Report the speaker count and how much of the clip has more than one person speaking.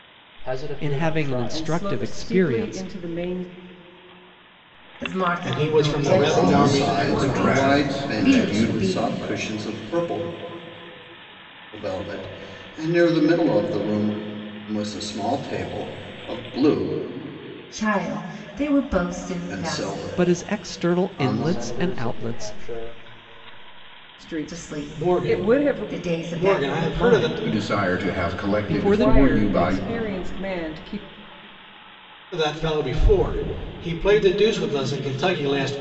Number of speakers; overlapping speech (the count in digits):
7, about 40%